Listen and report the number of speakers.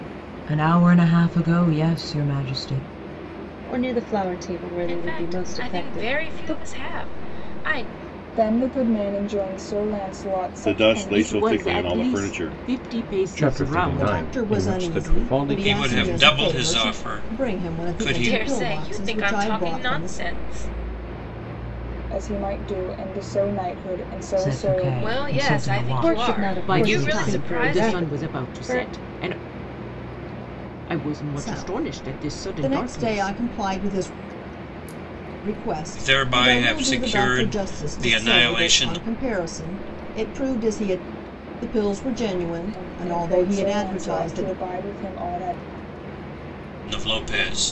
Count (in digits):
9